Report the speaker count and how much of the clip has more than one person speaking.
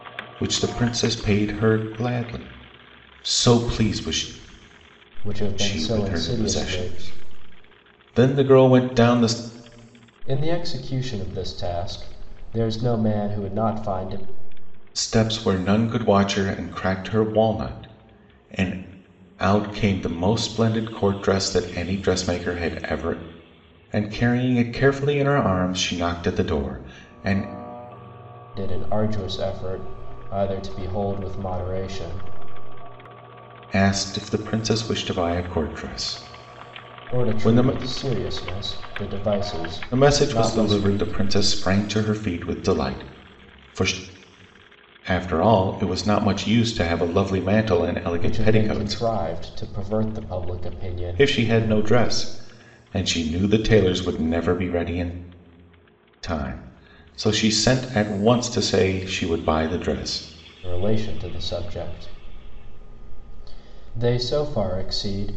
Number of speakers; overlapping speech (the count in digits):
2, about 7%